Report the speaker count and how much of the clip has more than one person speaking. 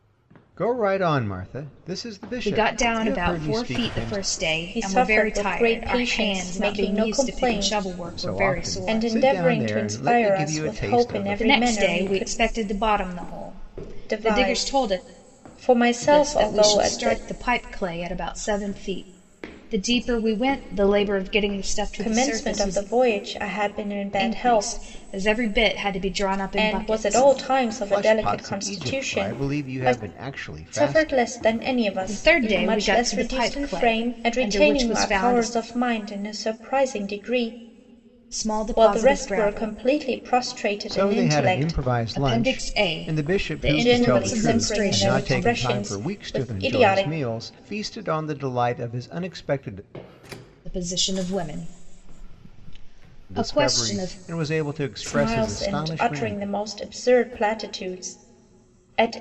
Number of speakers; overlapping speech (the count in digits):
3, about 49%